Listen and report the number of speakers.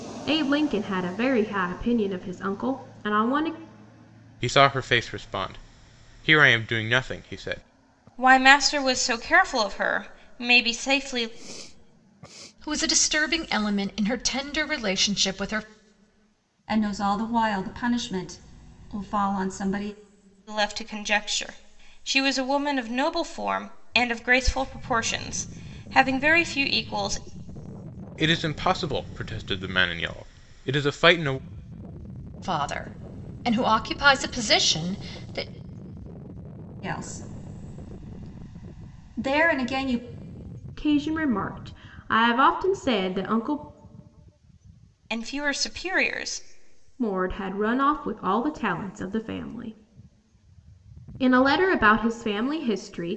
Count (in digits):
5